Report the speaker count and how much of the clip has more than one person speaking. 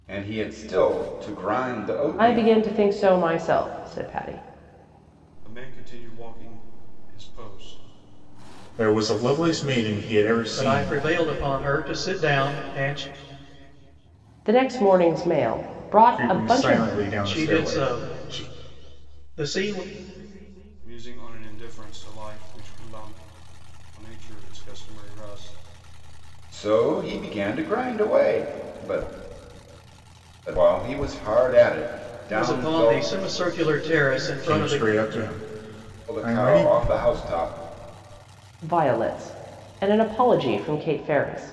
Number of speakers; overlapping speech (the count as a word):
five, about 12%